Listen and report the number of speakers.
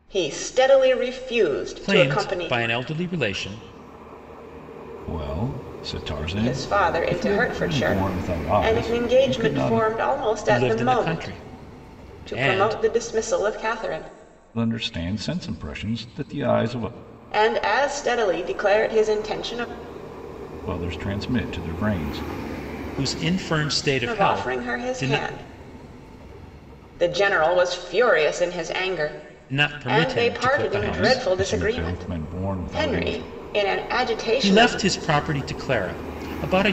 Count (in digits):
3